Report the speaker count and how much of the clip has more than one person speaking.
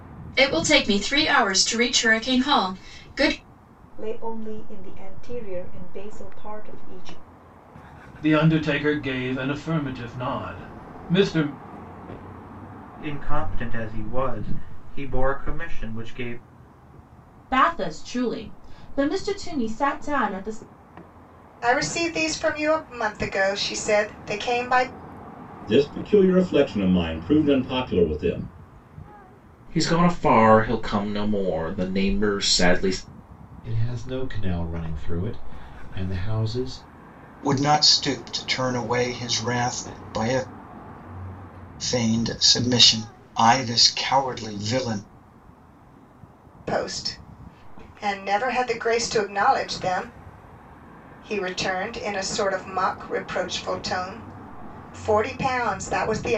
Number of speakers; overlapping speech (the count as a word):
ten, no overlap